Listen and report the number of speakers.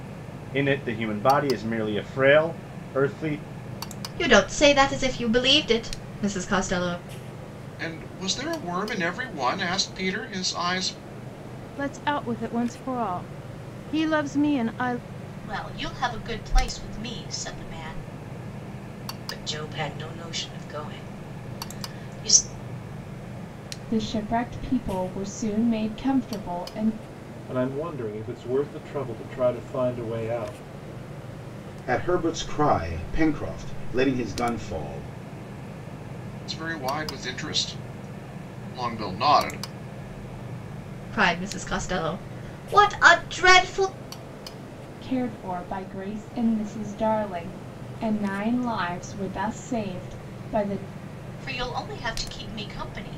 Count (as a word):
nine